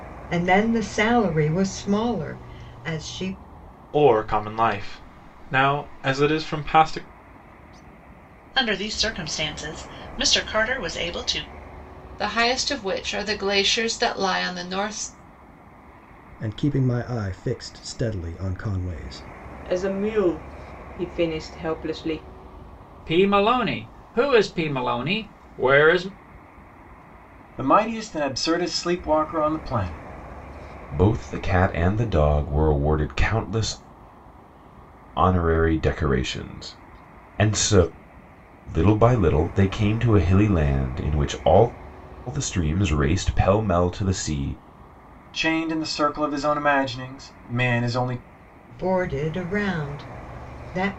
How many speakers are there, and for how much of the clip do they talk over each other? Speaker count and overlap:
9, no overlap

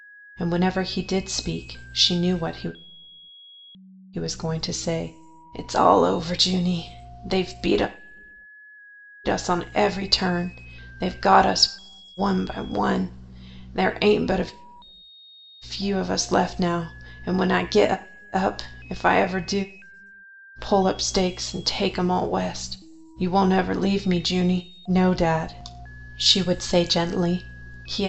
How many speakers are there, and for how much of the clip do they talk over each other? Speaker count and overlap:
1, no overlap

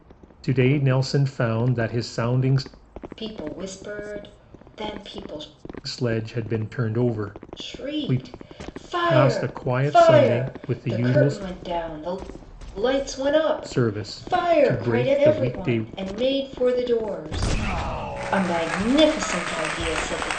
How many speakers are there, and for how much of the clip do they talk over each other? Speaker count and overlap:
2, about 25%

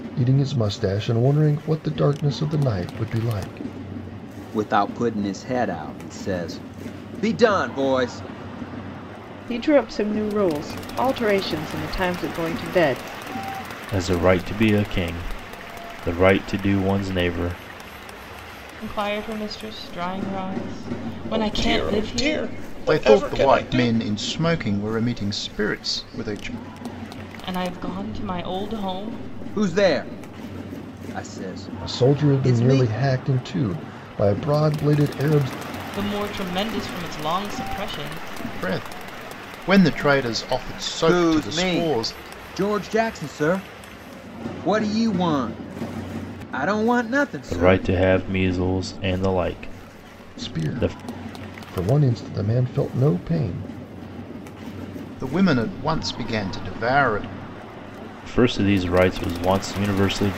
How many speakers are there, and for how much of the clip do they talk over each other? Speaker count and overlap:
7, about 9%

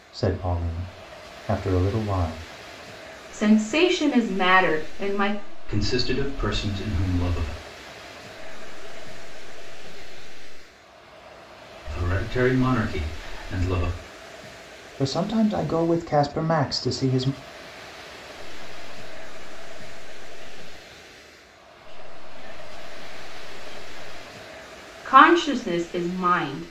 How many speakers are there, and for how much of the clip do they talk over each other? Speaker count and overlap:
4, about 7%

